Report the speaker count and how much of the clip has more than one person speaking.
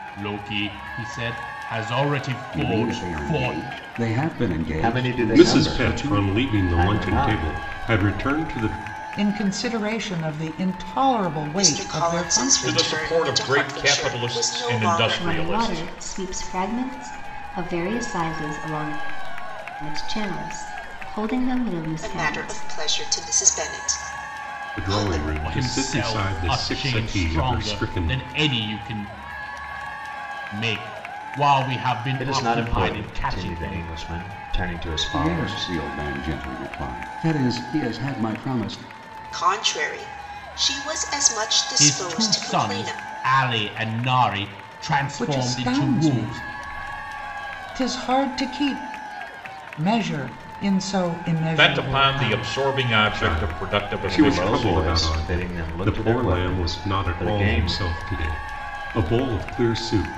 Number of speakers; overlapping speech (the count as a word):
eight, about 38%